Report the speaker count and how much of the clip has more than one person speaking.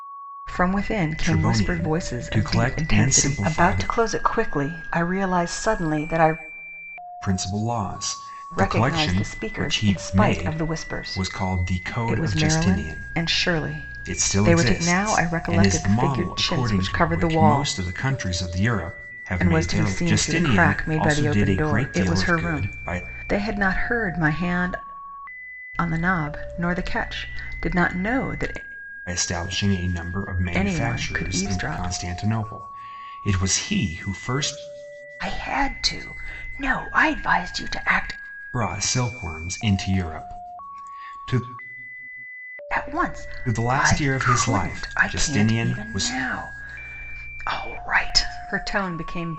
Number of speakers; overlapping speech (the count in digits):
2, about 36%